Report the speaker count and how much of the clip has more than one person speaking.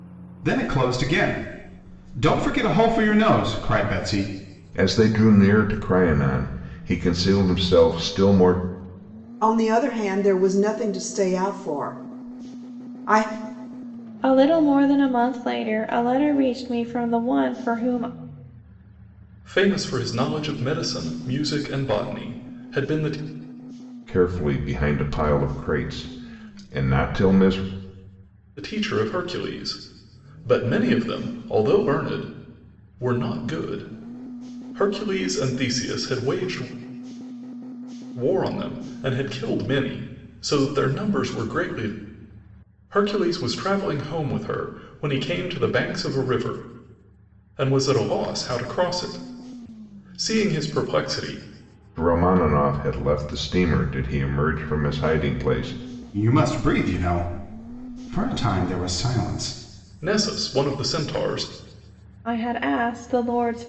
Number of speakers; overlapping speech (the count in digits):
5, no overlap